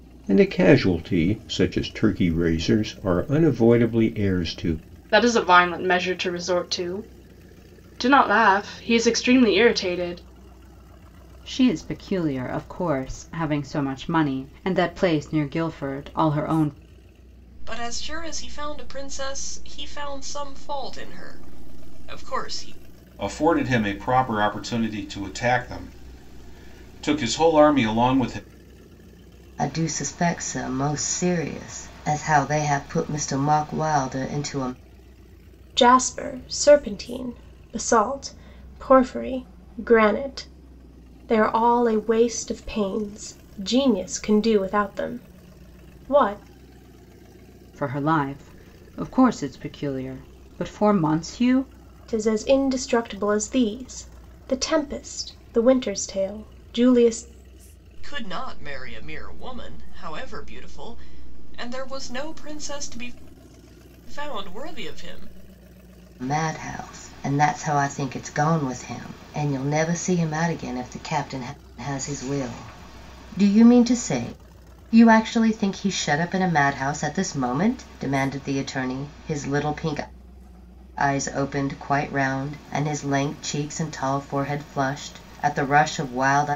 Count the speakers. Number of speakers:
seven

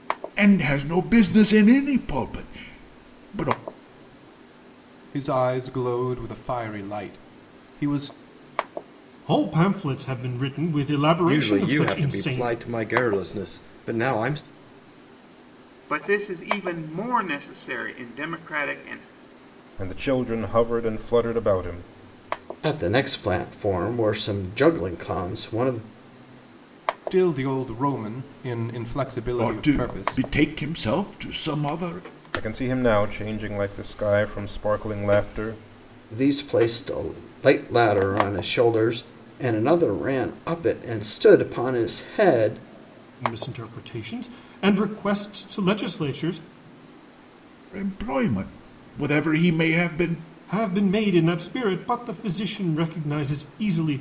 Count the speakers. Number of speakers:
seven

